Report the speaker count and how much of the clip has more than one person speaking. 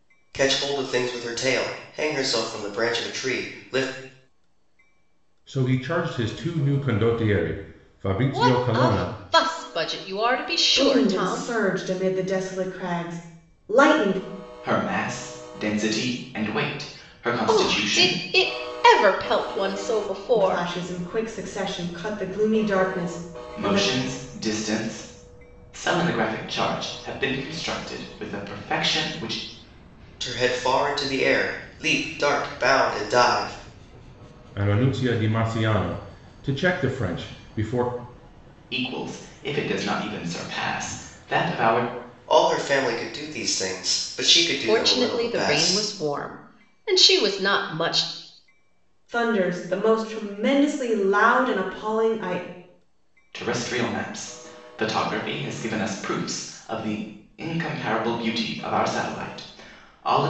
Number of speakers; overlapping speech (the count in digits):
5, about 7%